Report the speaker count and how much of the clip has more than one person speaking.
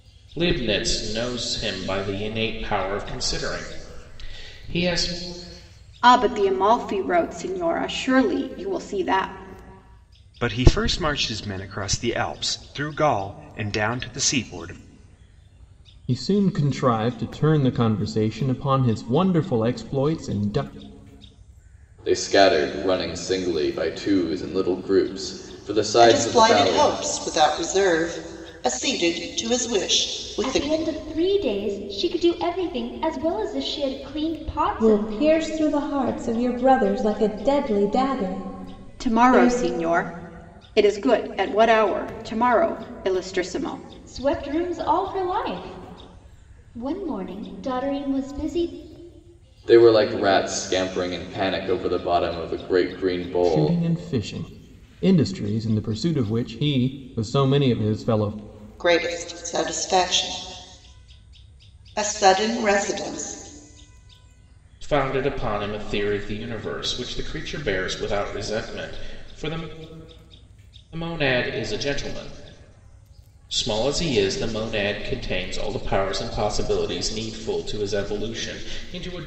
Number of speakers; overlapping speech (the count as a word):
eight, about 3%